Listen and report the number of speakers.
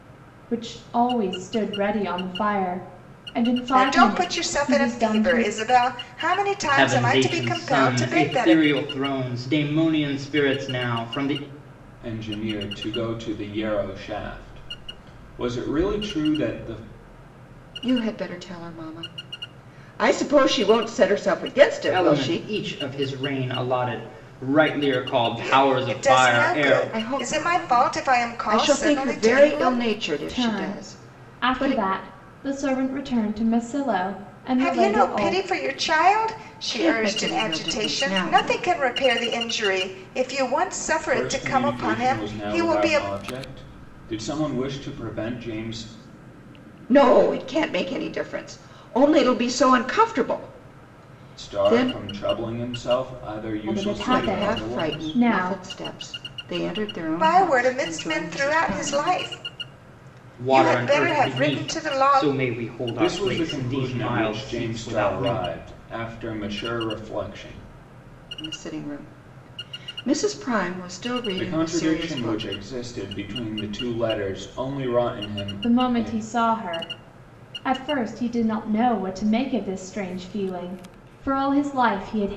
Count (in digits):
5